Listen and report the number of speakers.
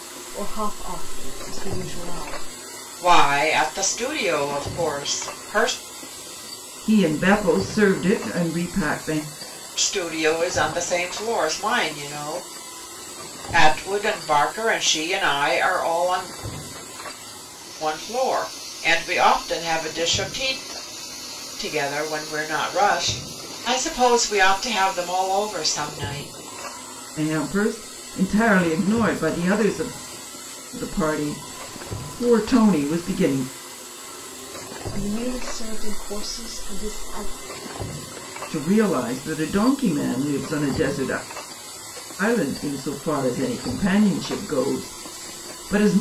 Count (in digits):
3